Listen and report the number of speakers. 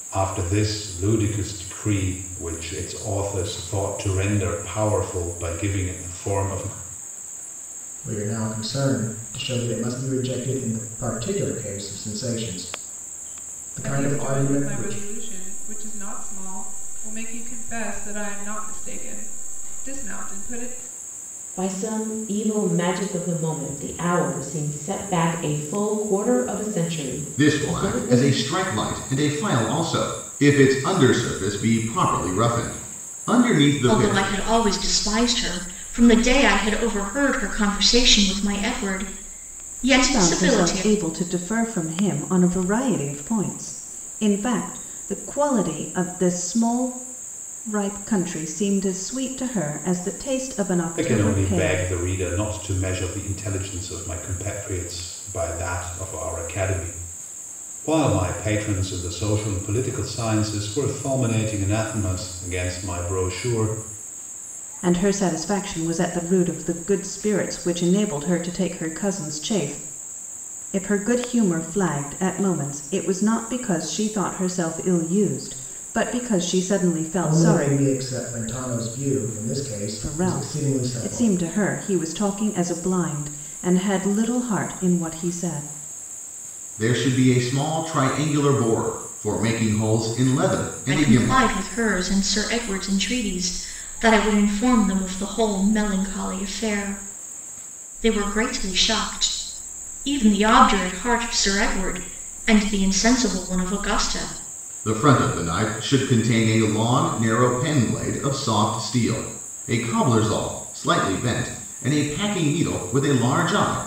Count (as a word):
seven